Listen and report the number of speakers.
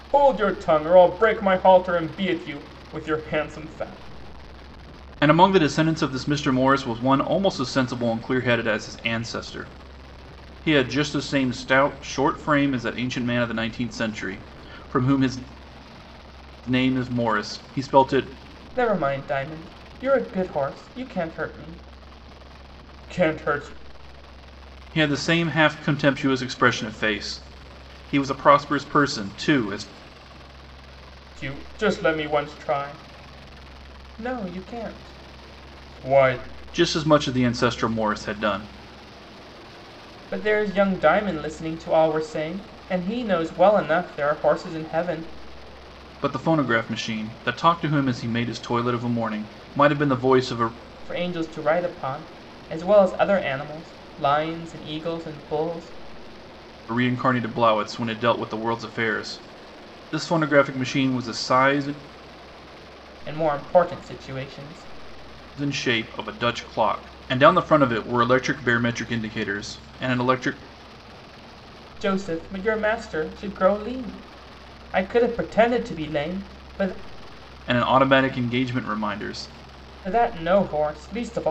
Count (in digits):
2